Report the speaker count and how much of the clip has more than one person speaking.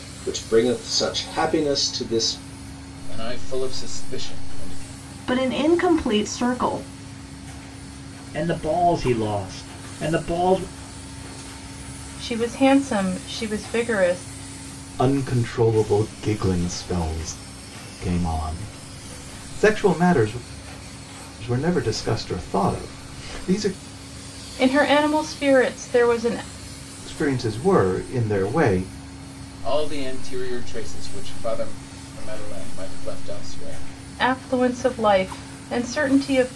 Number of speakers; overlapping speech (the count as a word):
six, no overlap